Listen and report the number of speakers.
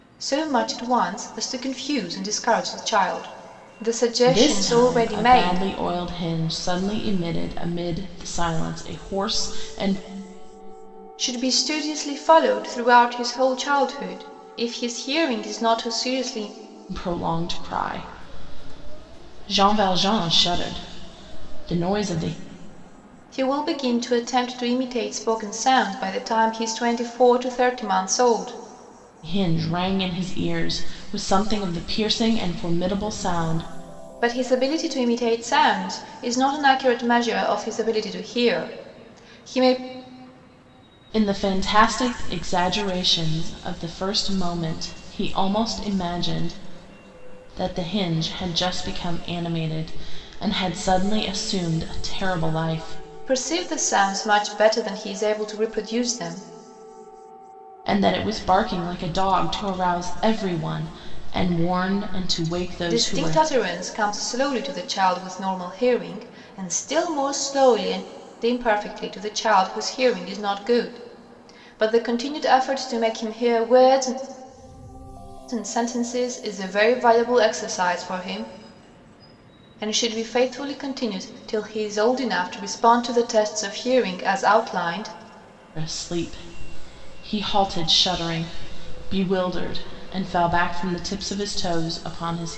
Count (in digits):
2